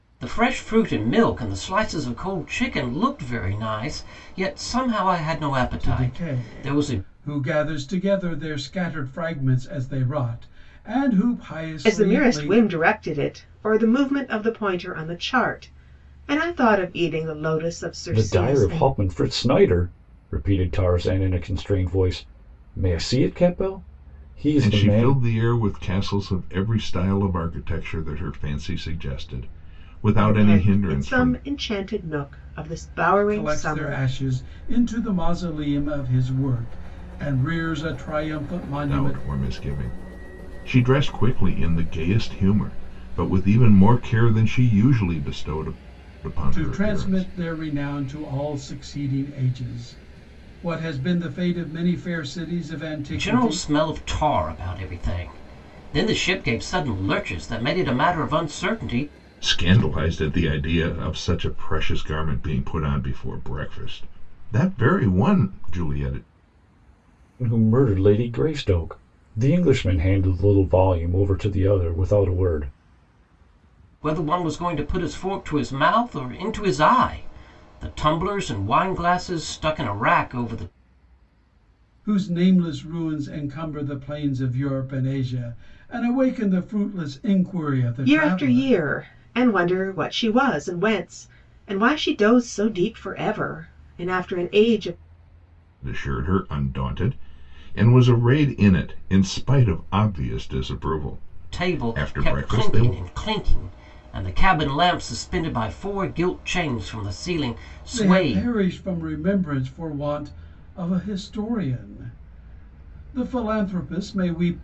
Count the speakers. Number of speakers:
5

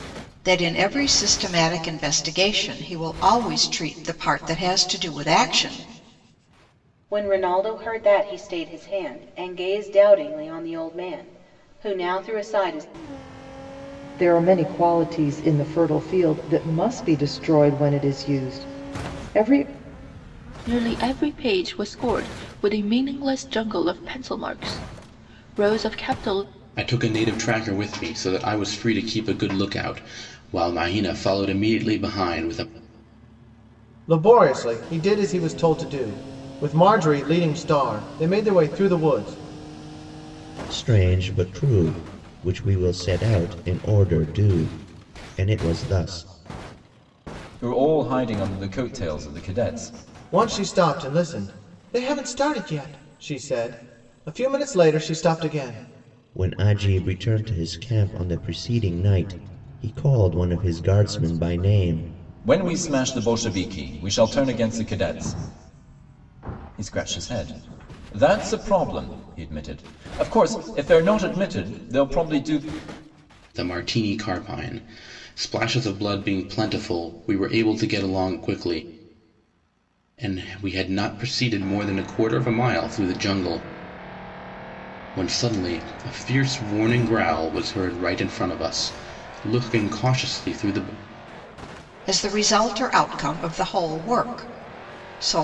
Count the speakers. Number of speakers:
8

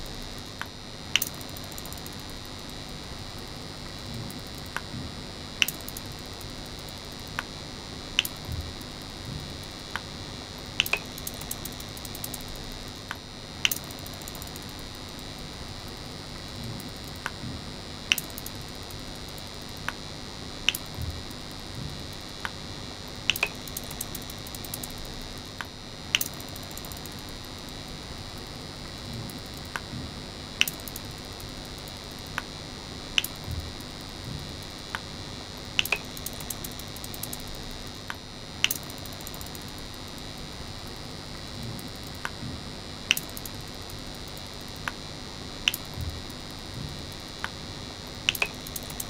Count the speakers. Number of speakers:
0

